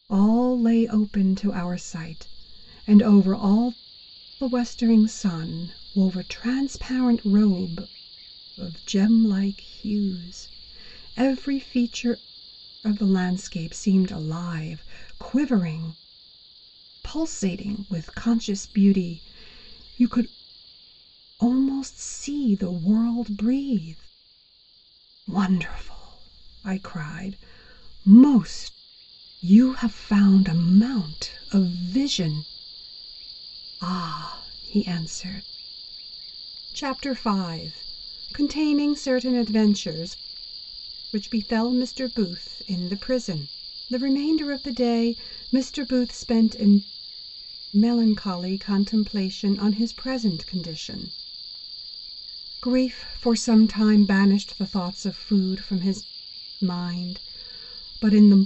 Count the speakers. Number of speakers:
1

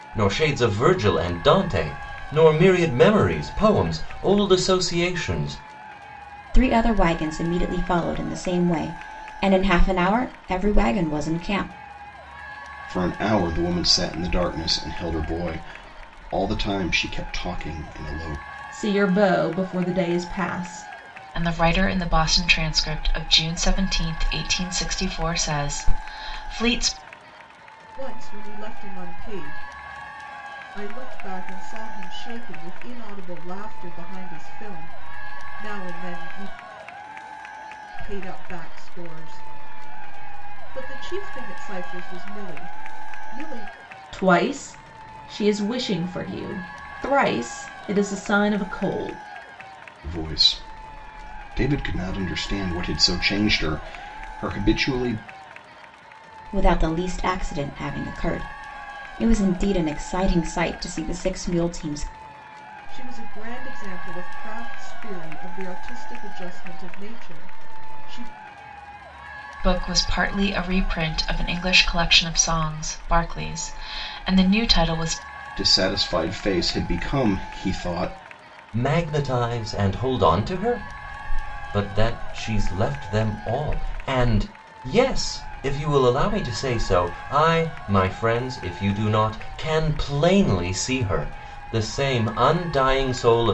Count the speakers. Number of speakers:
6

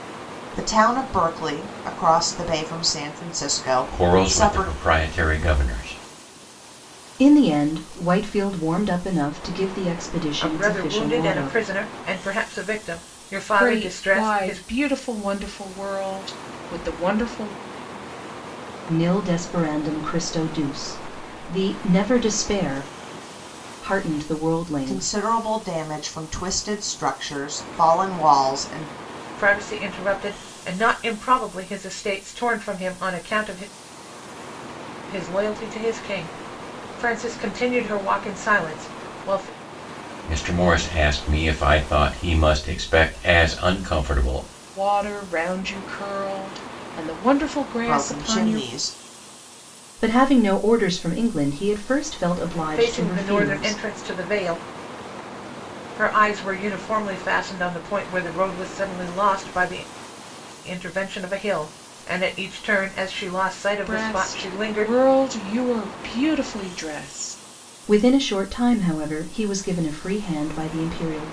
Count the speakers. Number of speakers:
5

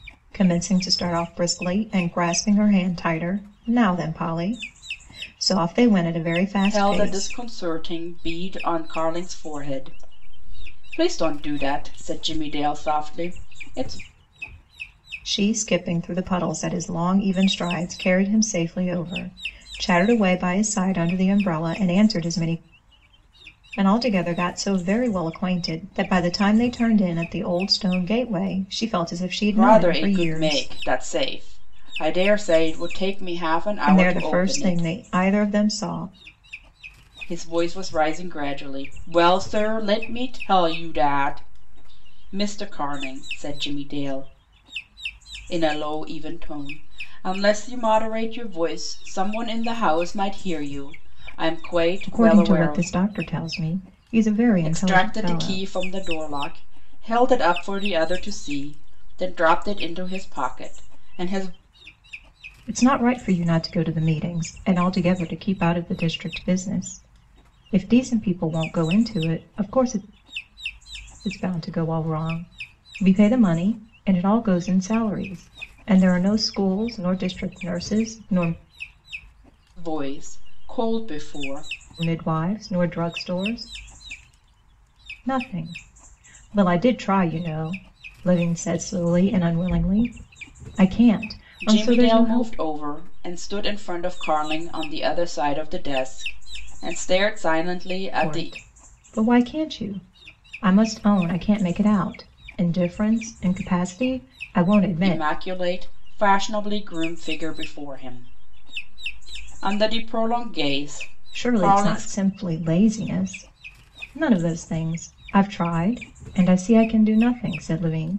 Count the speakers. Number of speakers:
2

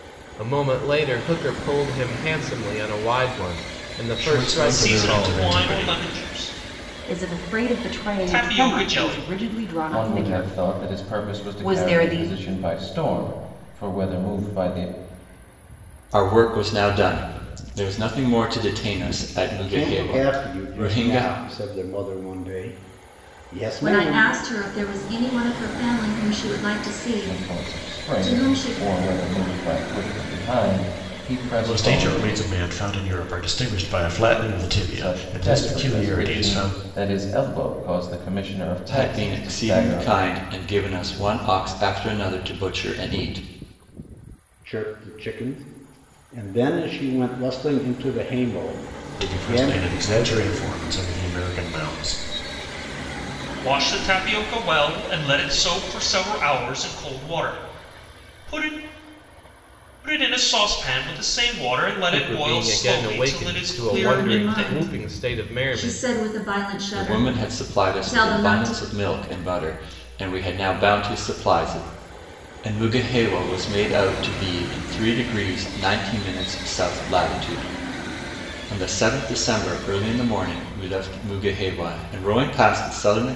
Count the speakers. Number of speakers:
8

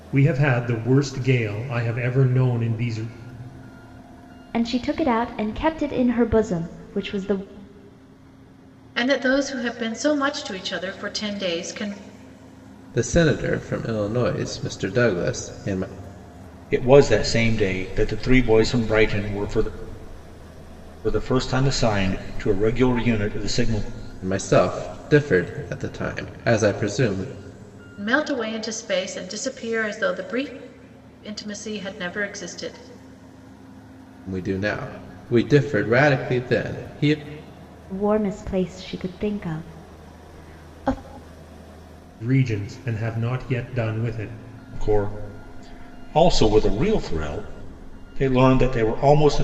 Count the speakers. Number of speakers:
5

